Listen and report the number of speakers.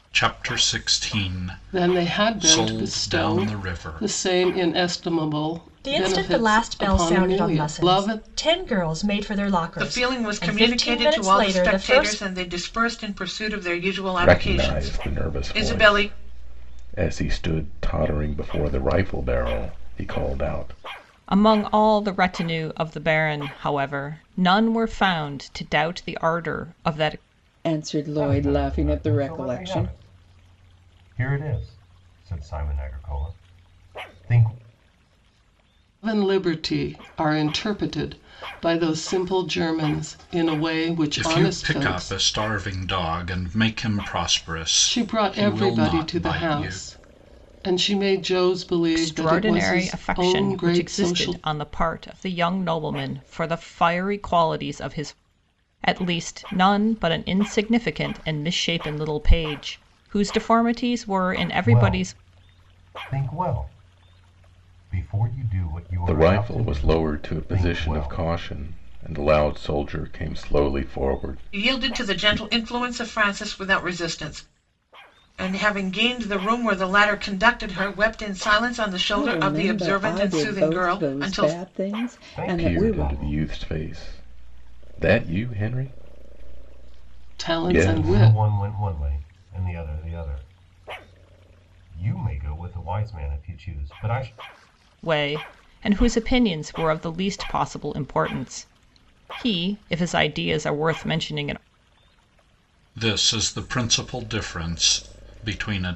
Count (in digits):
8